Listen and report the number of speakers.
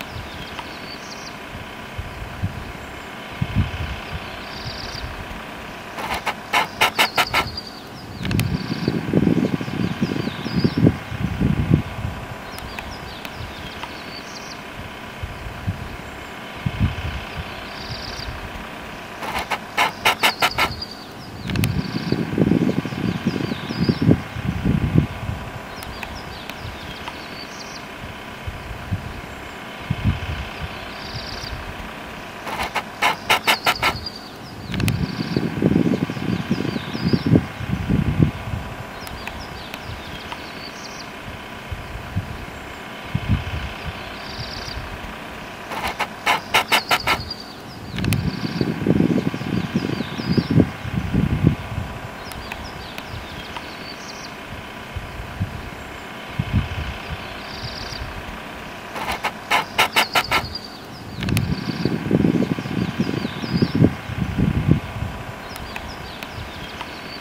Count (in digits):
0